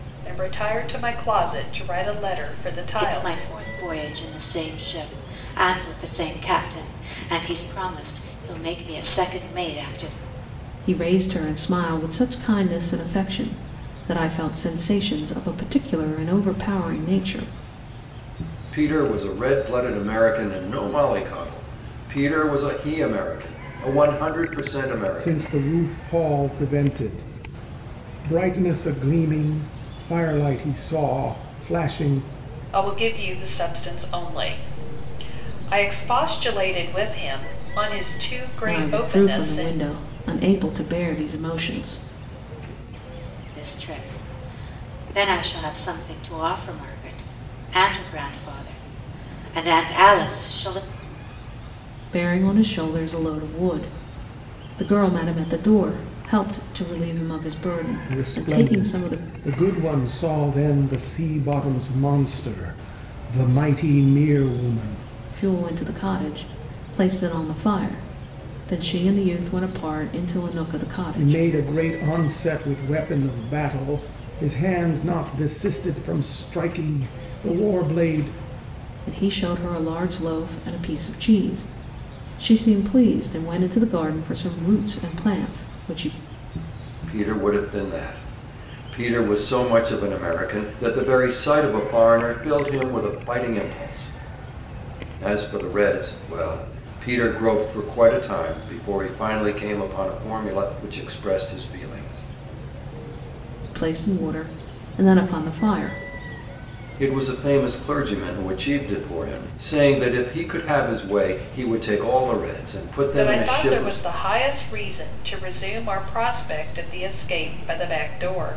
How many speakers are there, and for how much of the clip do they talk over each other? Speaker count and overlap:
5, about 4%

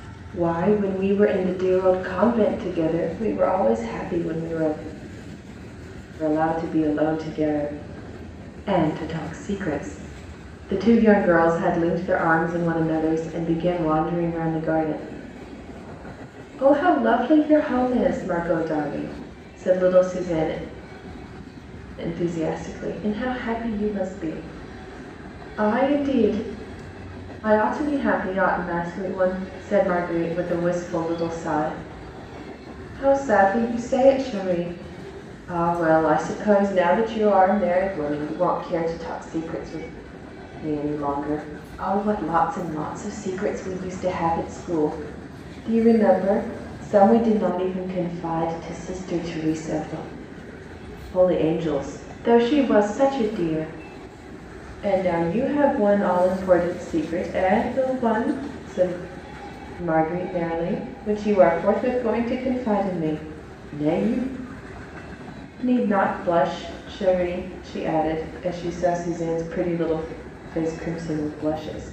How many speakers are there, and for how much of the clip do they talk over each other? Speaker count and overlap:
1, no overlap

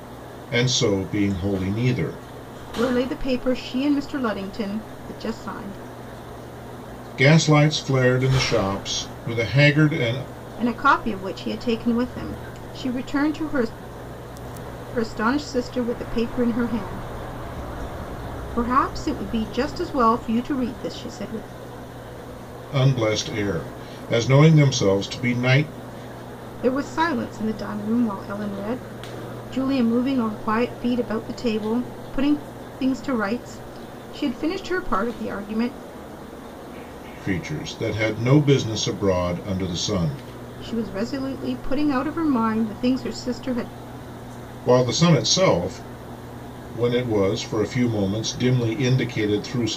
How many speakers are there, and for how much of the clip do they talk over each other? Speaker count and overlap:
2, no overlap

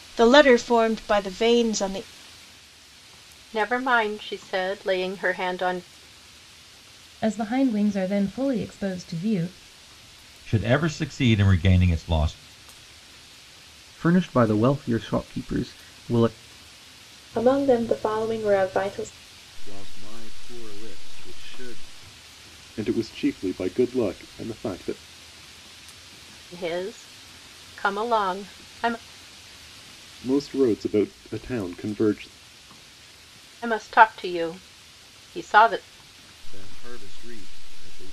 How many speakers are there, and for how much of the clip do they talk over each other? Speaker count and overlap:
8, no overlap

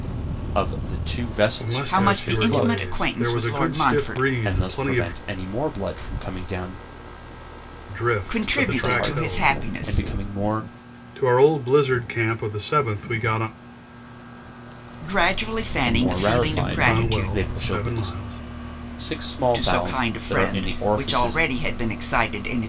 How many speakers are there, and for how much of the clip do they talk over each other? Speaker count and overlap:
3, about 43%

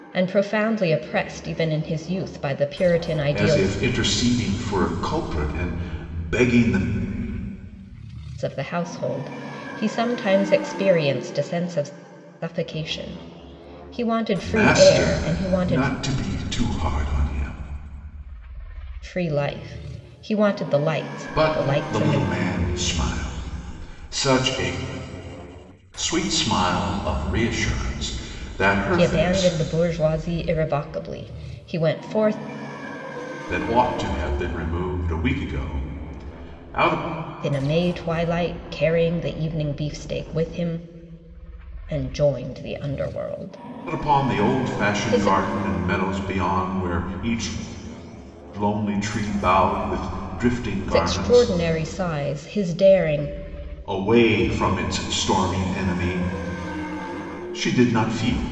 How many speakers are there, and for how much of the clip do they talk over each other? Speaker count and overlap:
2, about 10%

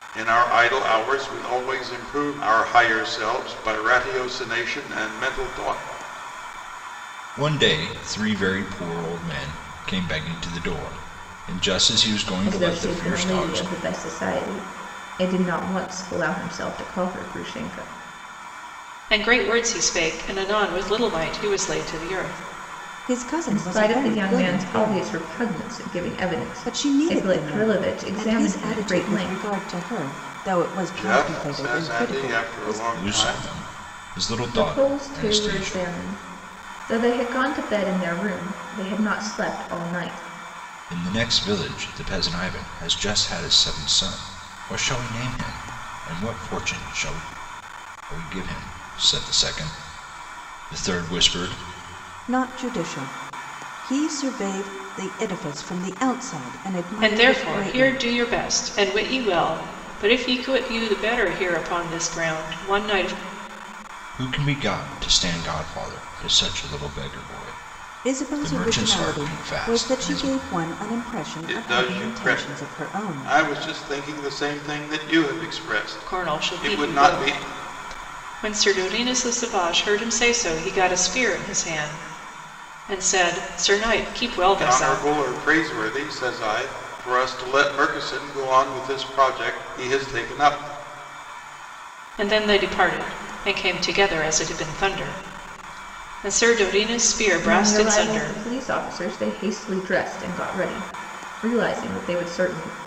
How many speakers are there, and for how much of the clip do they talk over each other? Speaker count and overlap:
5, about 17%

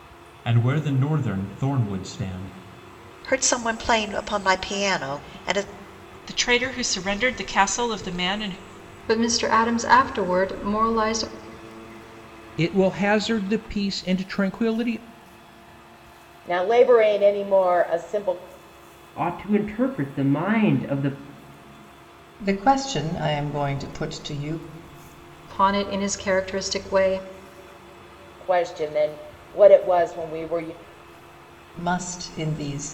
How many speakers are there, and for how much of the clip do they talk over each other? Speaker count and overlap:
8, no overlap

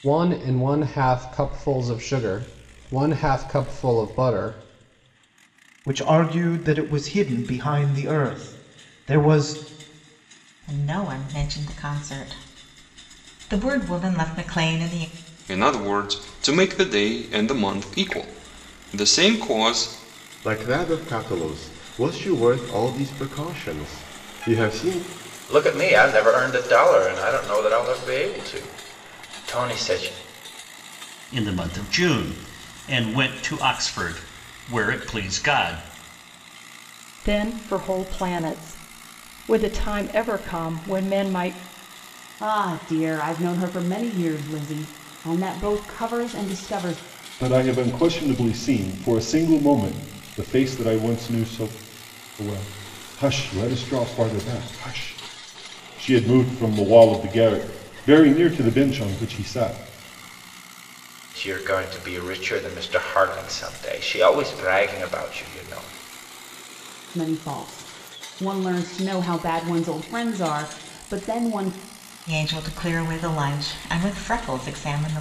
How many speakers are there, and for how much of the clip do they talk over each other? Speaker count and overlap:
10, no overlap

